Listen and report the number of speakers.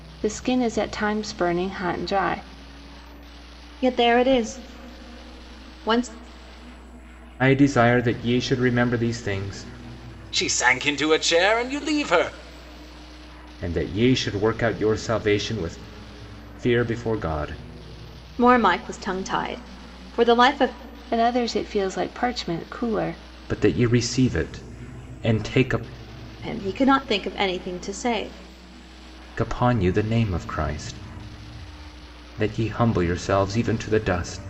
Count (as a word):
four